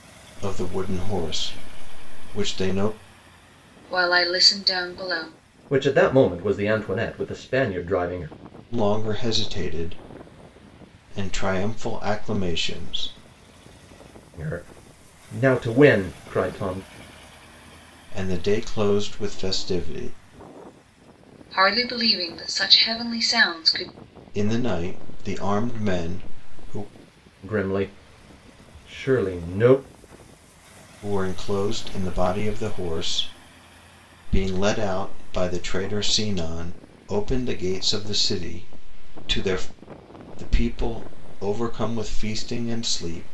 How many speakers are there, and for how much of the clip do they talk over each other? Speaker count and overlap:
3, no overlap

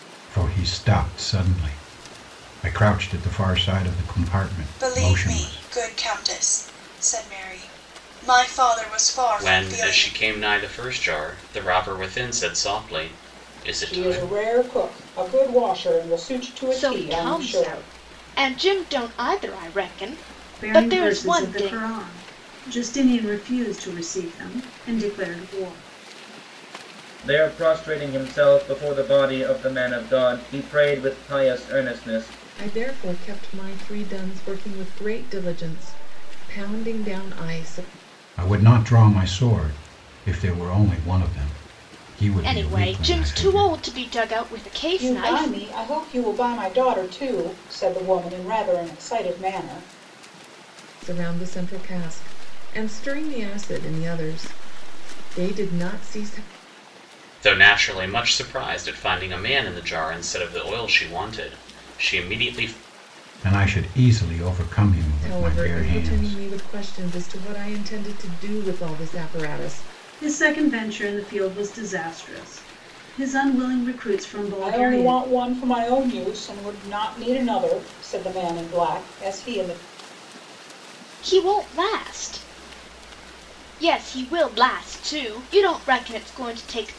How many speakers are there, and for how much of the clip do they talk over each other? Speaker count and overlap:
8, about 10%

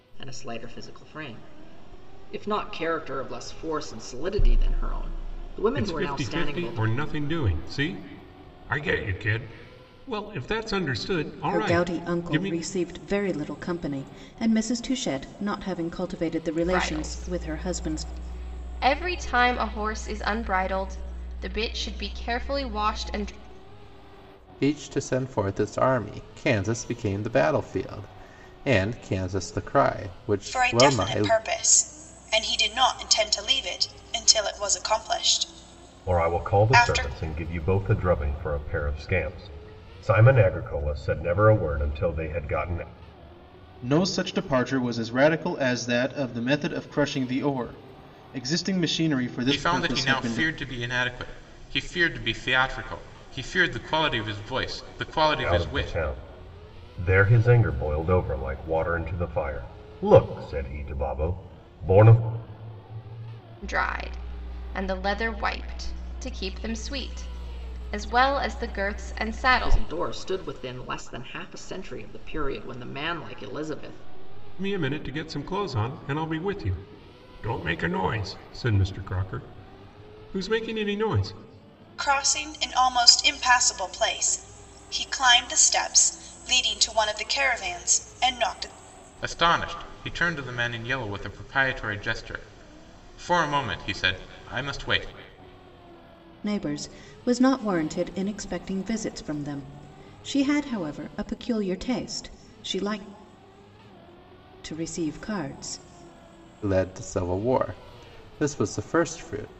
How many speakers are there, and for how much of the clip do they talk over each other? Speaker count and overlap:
9, about 7%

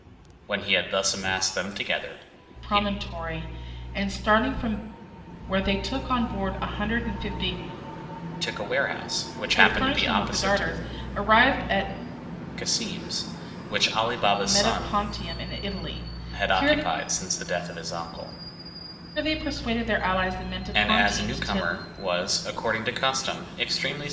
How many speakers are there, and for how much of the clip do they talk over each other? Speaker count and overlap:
2, about 15%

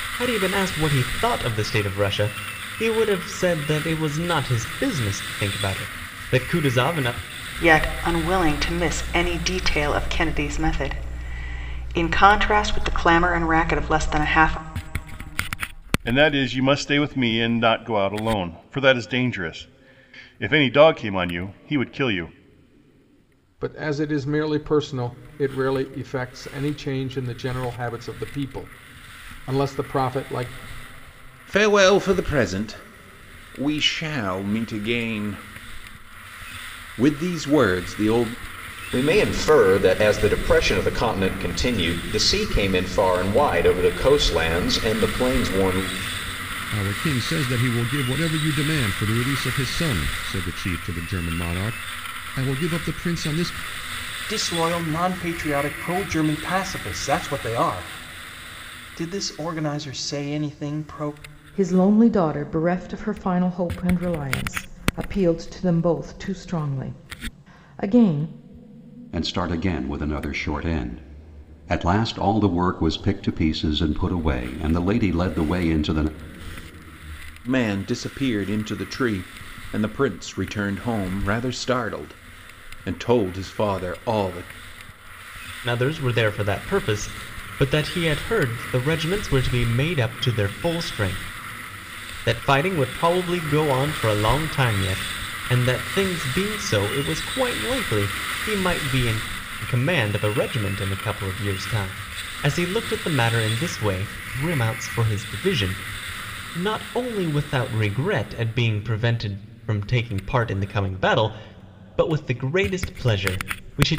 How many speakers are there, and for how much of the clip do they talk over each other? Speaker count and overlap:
10, no overlap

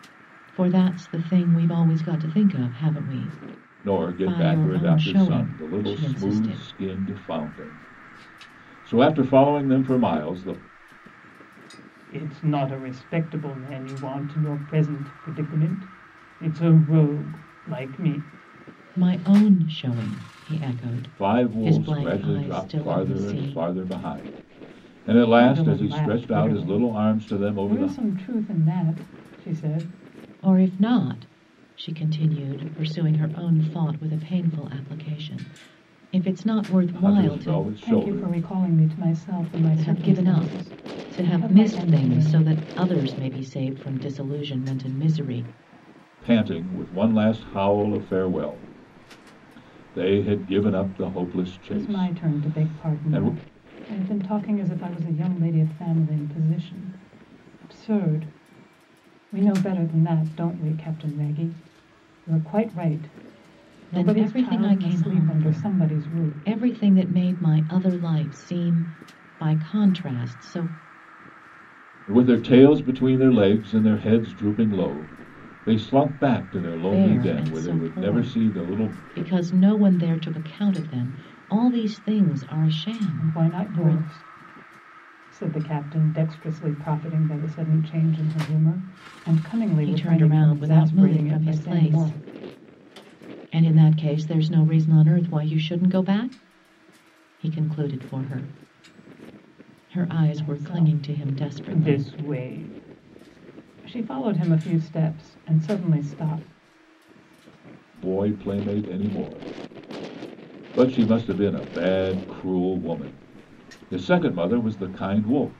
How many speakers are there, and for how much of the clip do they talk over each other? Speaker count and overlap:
3, about 20%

